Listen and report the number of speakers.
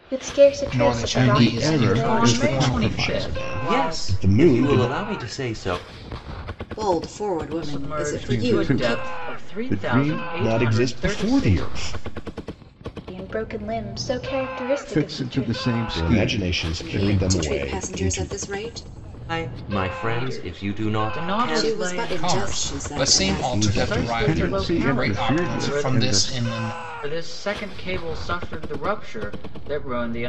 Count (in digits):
7